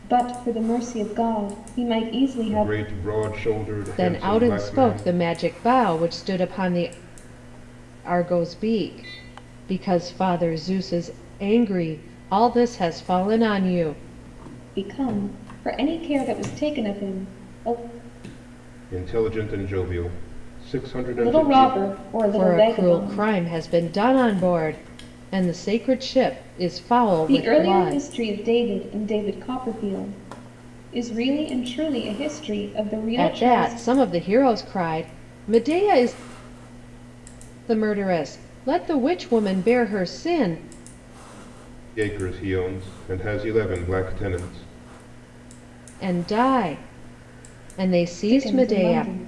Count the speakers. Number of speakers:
3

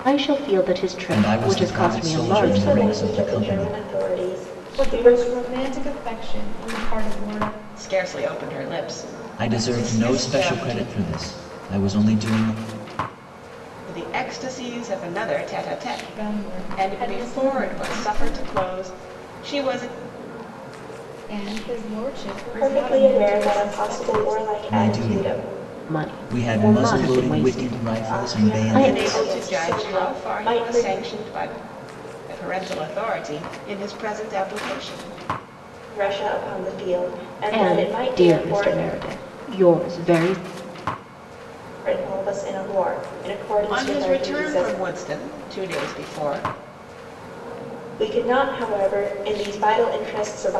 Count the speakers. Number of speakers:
5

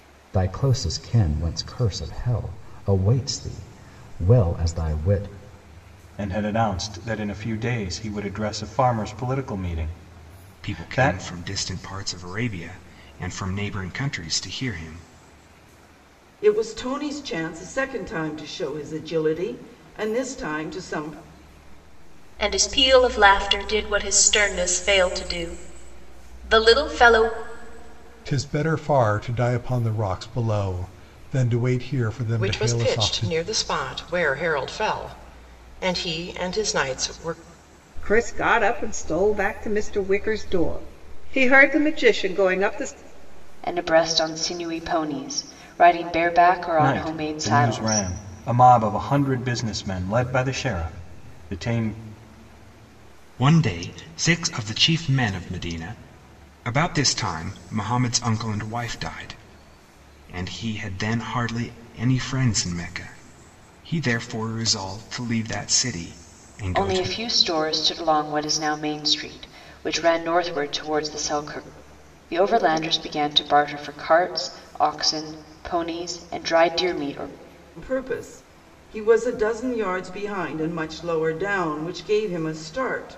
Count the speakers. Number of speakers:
9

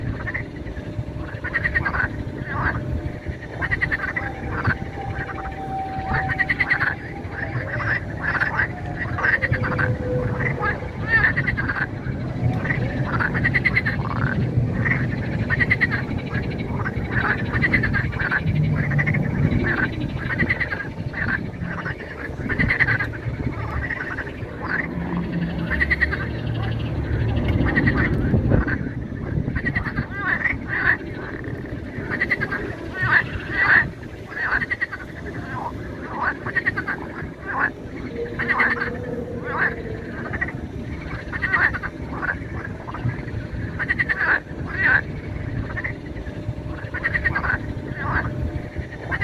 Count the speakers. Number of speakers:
0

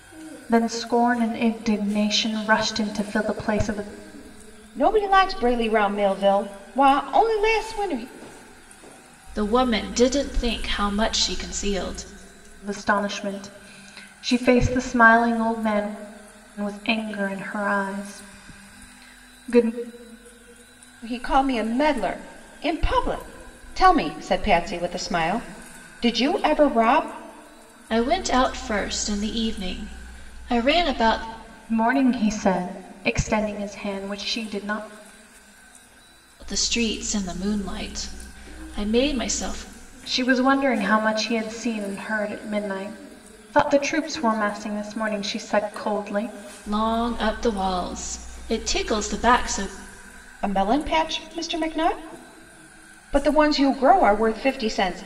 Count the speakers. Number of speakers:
3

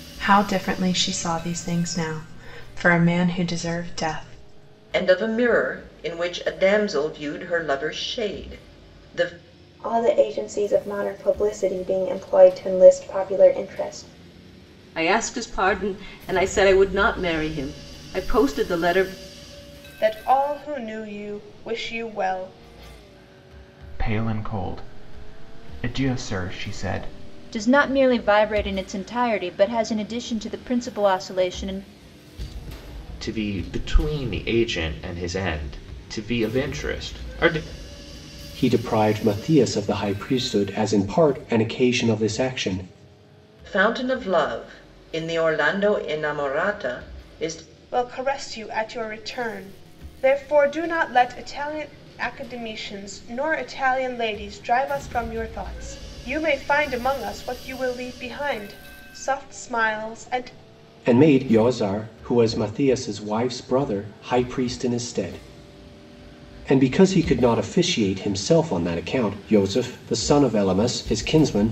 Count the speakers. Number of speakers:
9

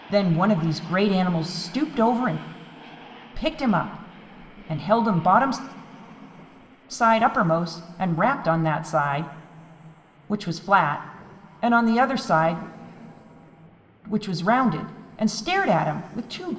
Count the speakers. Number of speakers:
1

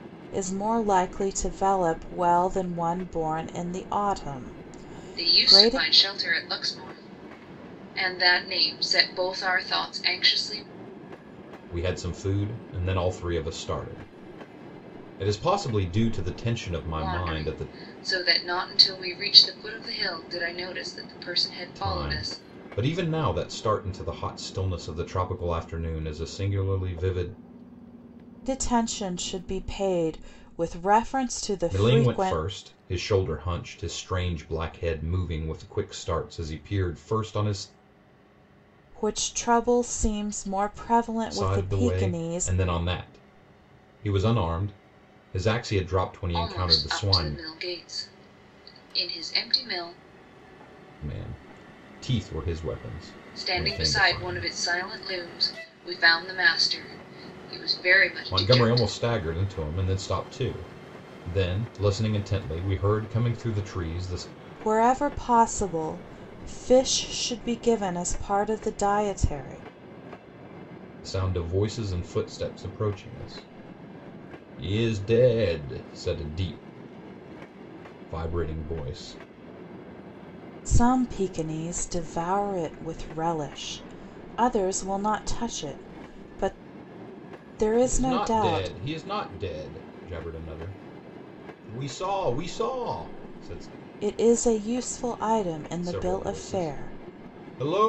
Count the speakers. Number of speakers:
3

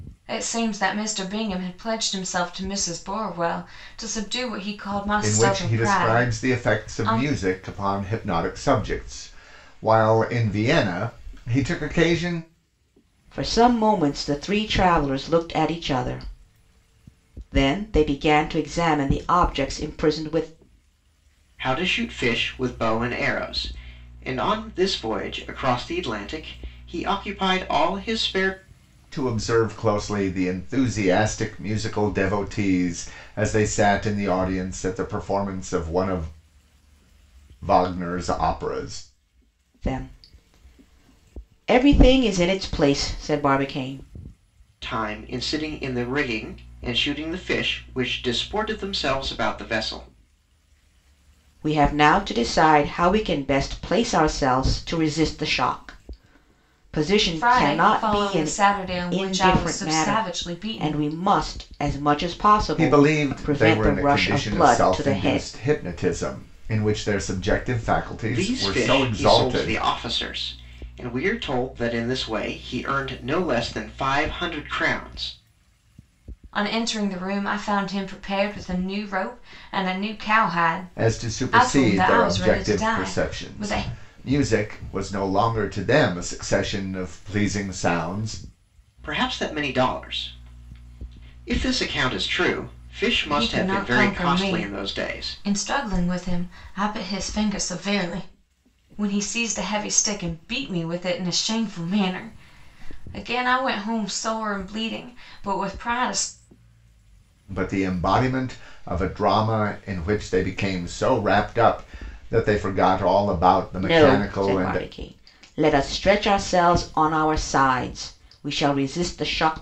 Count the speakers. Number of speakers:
4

